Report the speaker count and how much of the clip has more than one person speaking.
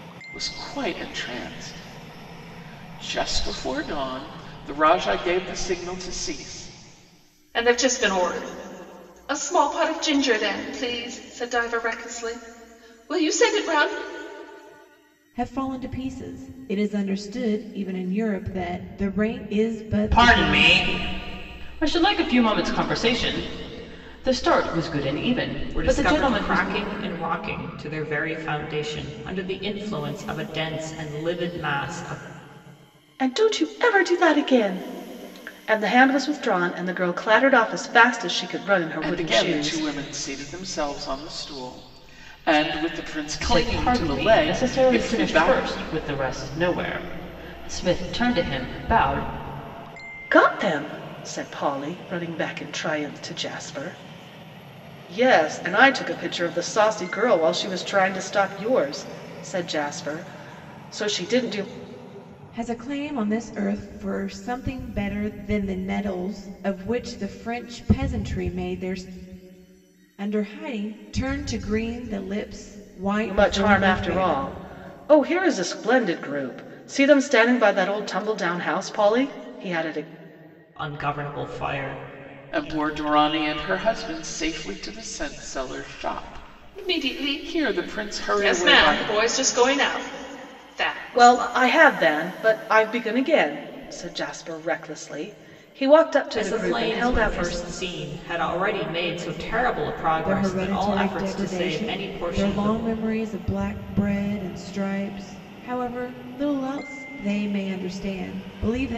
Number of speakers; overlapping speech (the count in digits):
6, about 12%